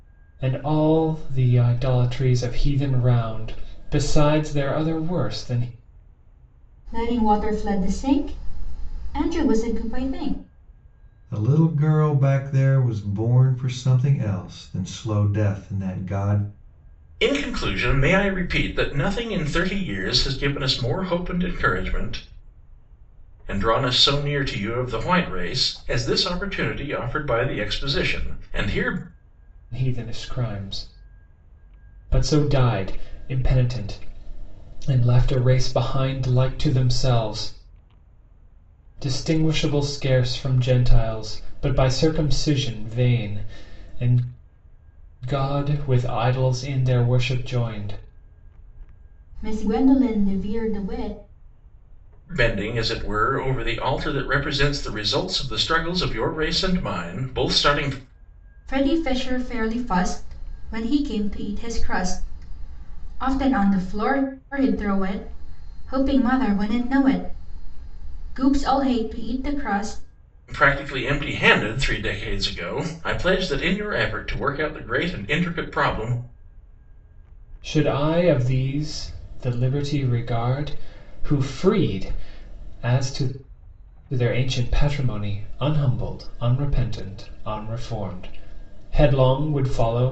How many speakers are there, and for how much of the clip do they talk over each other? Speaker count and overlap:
4, no overlap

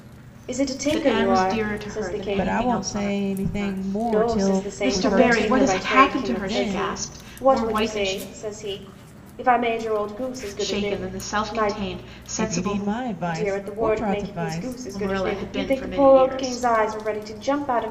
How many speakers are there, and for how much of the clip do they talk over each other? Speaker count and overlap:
3, about 66%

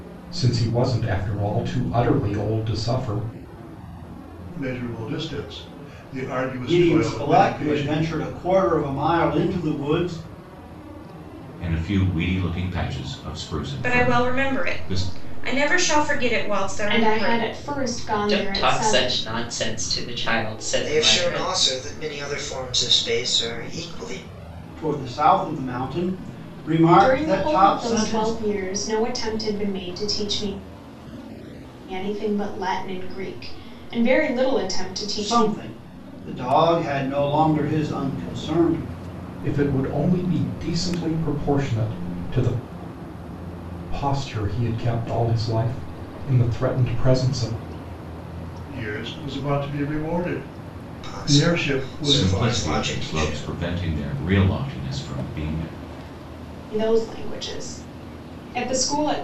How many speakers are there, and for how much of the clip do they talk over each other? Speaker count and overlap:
8, about 16%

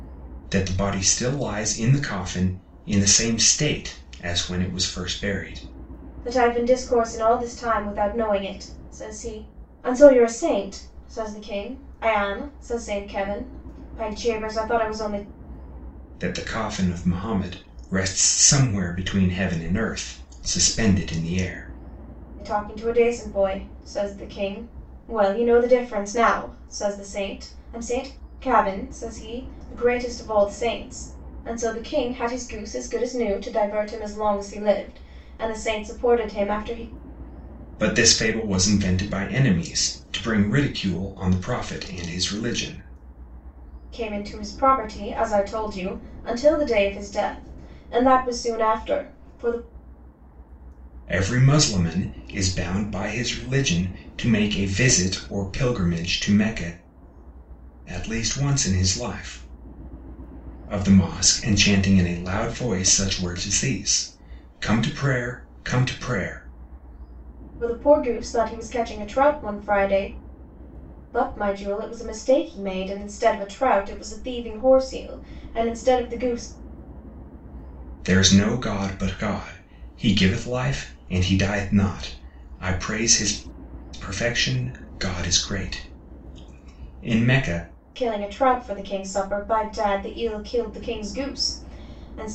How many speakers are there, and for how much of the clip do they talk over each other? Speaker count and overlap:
2, no overlap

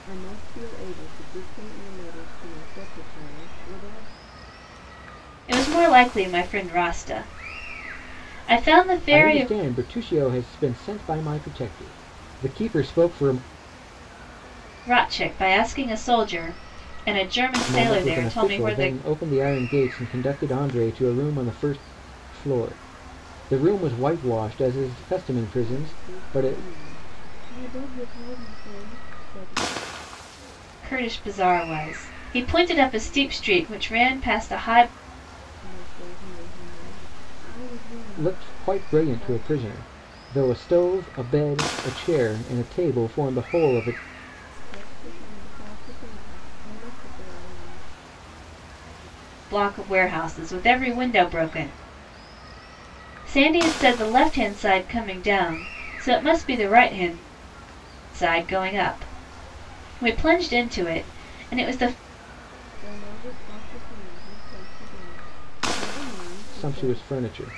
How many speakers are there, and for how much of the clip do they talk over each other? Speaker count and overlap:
3, about 7%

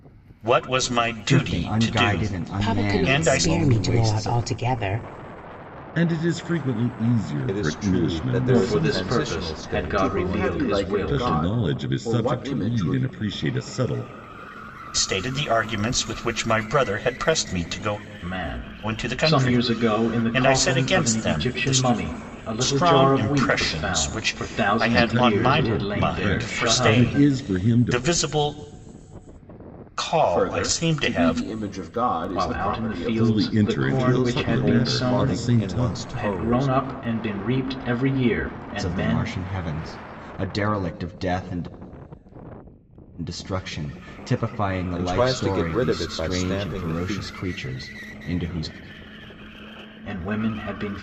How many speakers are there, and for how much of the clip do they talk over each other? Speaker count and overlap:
7, about 51%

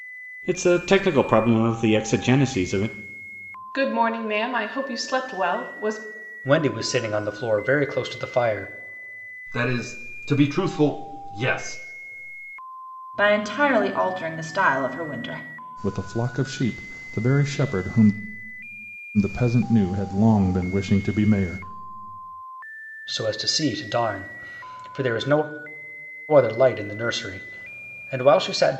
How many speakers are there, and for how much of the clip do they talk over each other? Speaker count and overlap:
6, no overlap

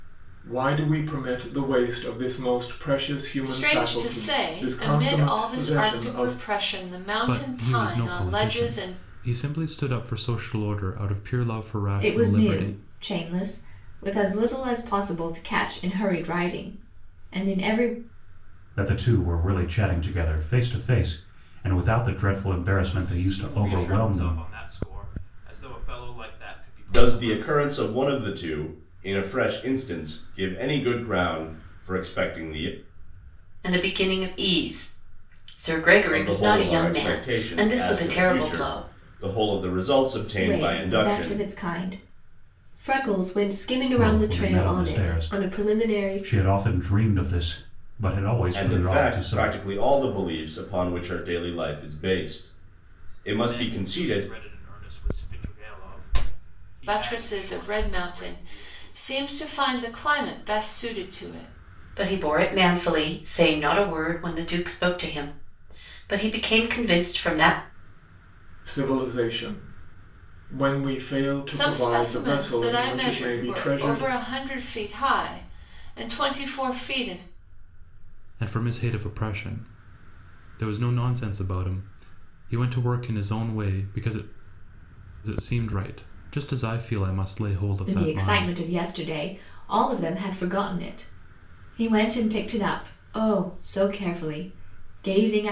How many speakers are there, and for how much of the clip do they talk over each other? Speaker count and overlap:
8, about 23%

